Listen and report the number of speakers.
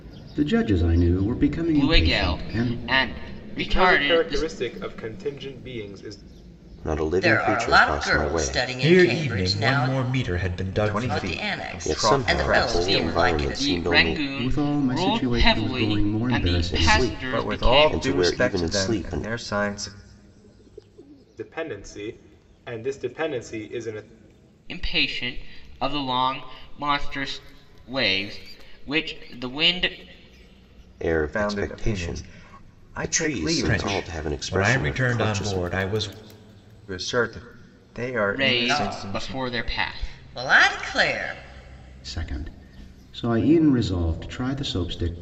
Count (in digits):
7